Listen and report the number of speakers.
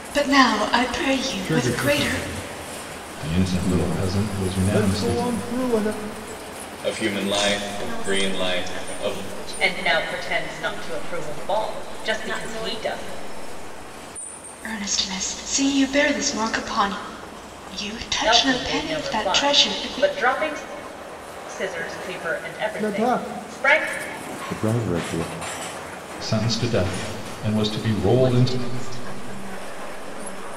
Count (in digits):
7